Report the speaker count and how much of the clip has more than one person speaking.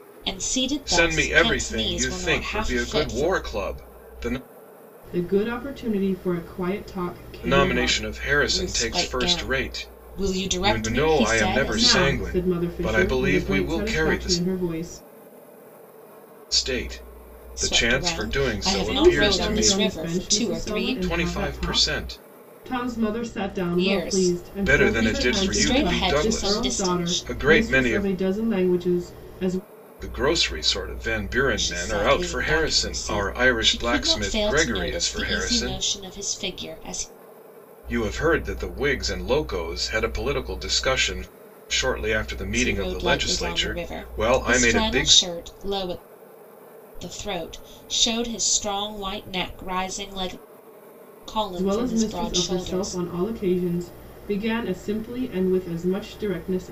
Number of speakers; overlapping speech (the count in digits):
3, about 46%